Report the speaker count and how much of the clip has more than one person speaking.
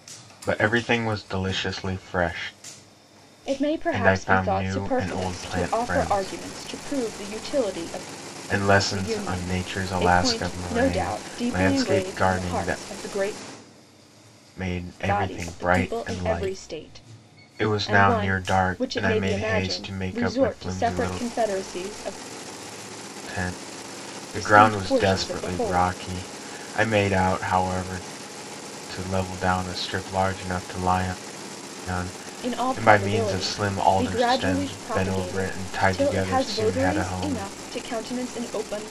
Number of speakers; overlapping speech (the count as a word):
two, about 47%